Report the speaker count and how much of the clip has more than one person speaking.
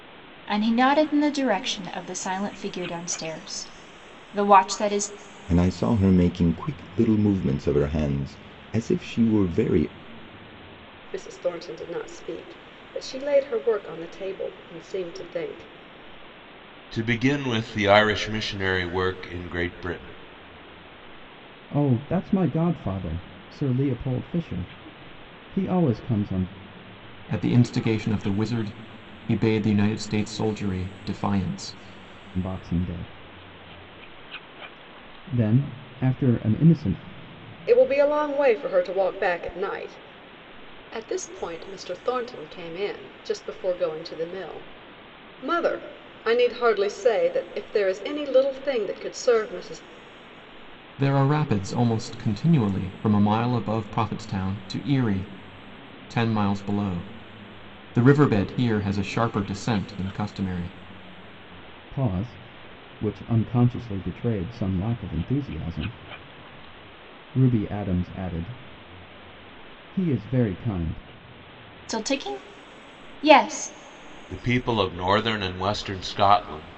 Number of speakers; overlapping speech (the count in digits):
6, no overlap